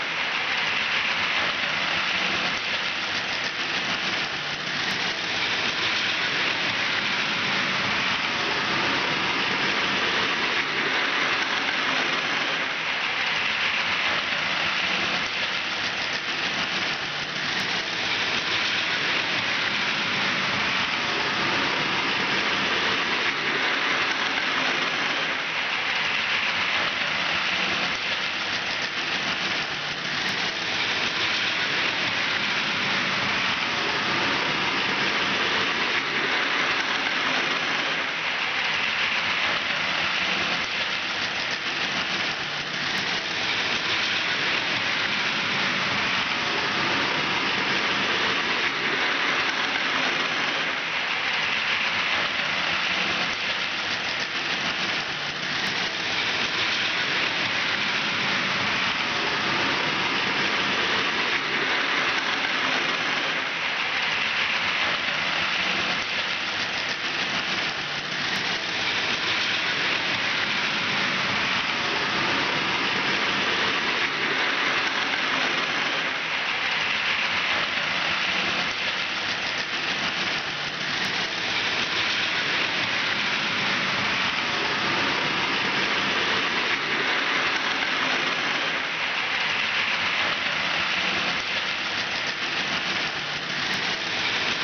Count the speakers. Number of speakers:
0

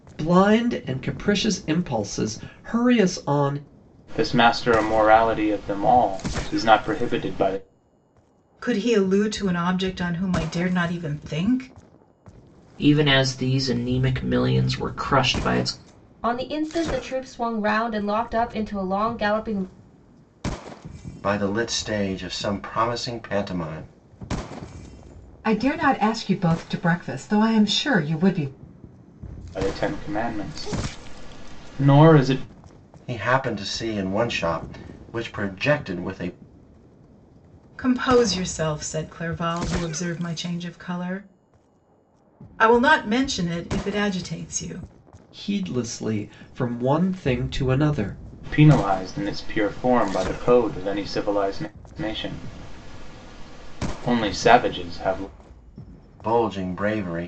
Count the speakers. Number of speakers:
7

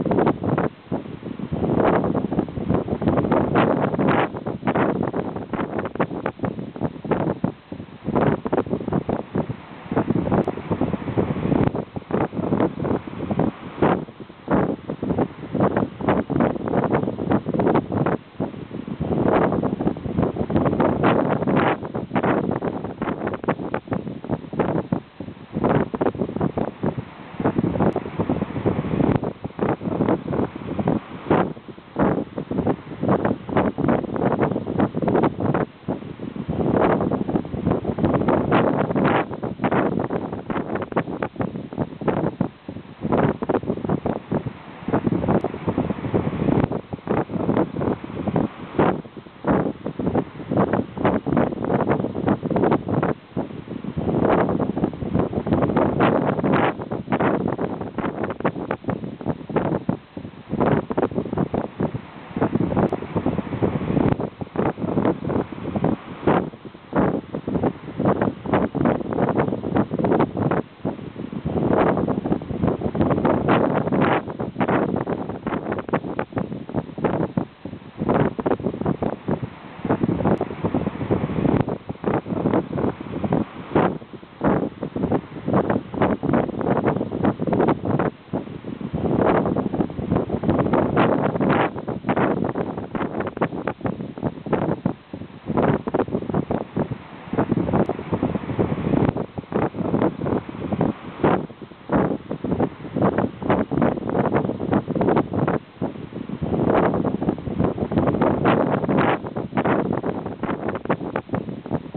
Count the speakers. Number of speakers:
0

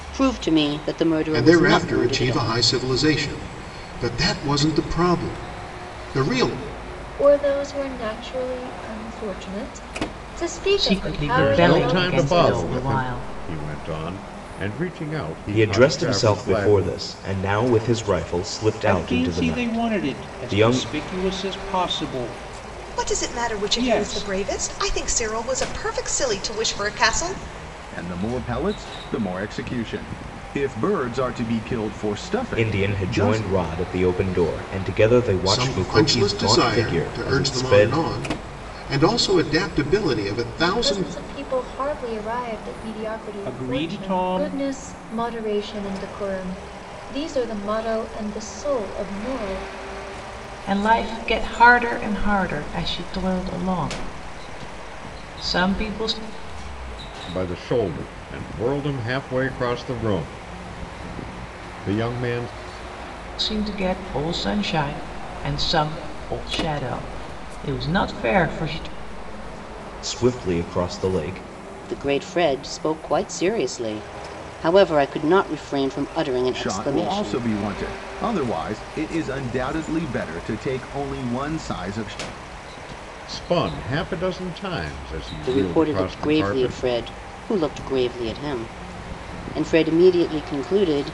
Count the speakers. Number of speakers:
9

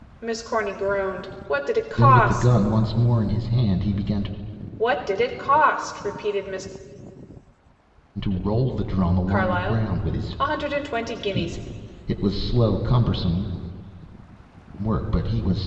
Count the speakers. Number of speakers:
2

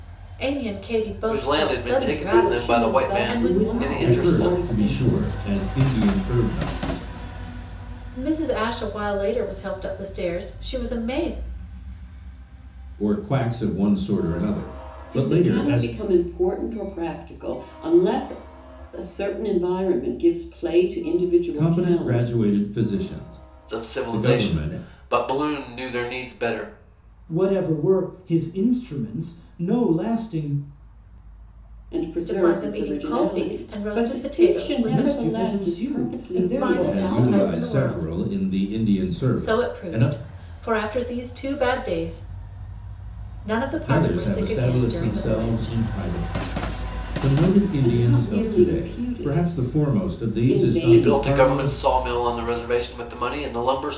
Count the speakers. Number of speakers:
5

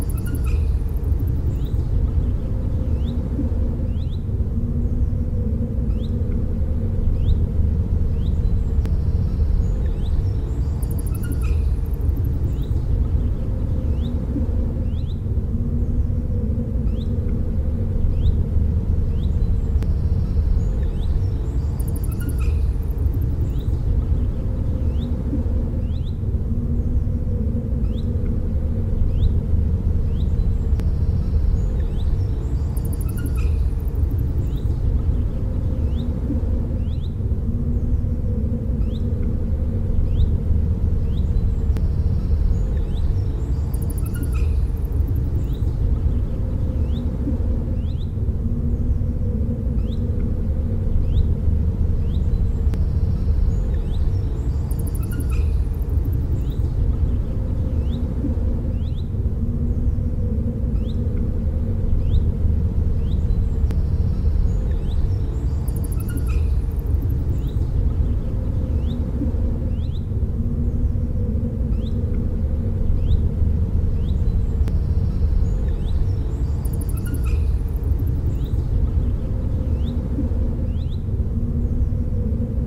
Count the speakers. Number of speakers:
0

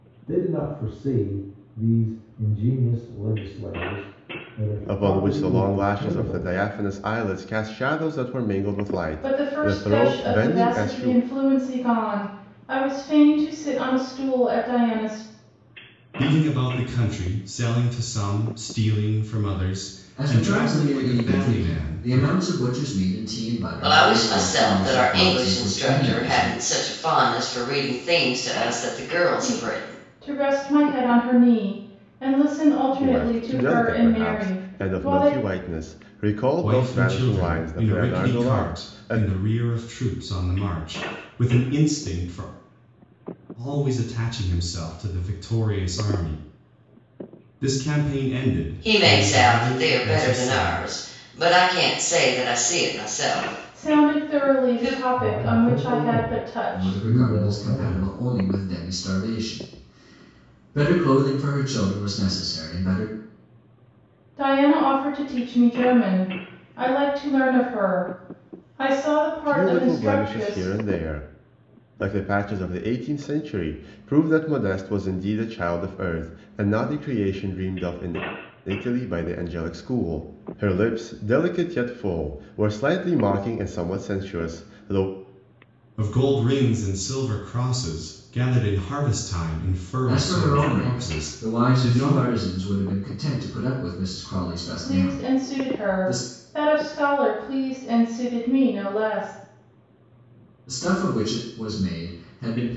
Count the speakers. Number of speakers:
6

